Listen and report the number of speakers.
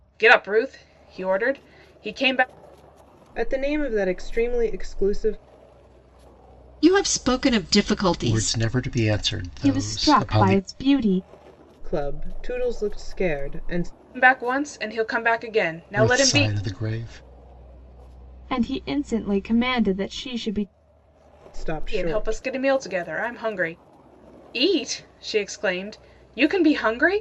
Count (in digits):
5